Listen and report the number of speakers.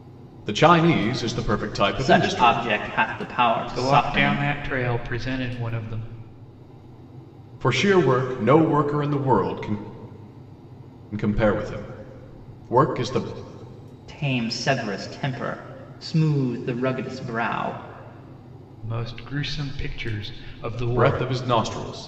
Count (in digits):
3